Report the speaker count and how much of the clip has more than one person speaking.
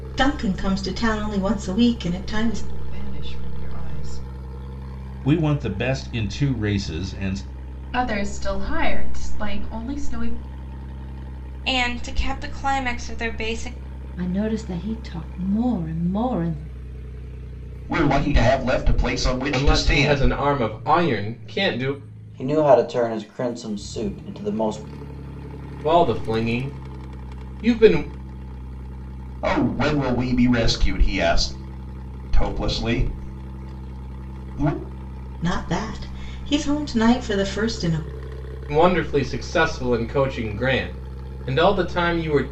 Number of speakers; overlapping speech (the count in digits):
9, about 3%